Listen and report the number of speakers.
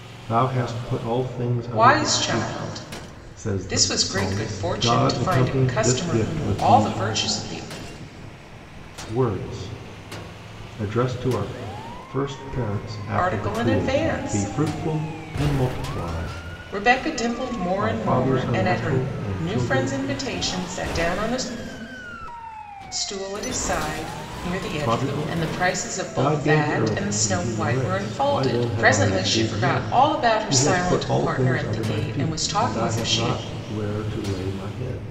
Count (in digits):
2